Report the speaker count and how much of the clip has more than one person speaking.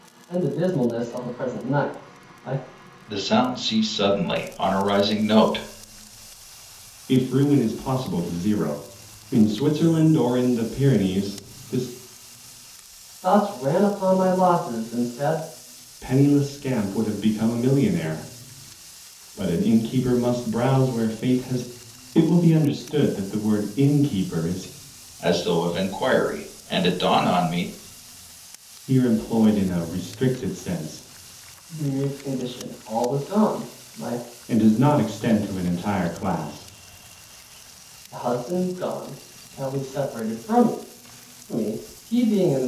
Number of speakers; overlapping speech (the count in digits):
3, no overlap